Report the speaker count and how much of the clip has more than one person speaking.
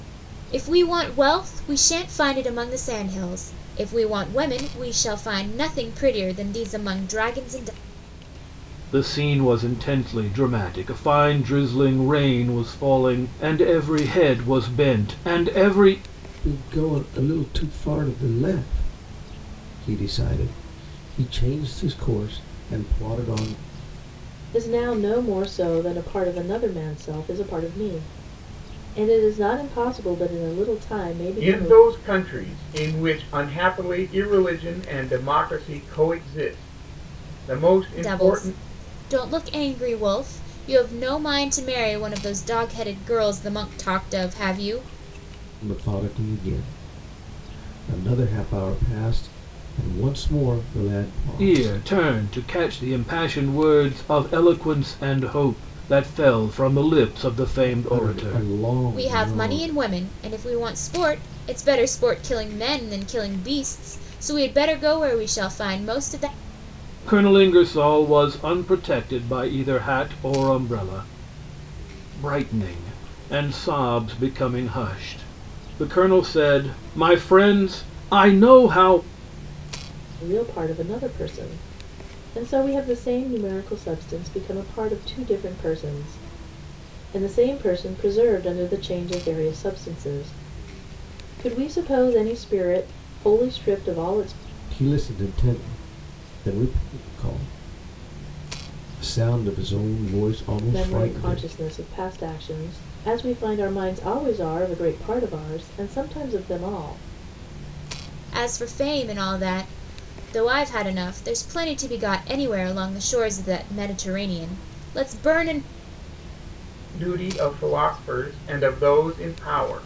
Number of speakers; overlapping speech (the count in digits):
5, about 4%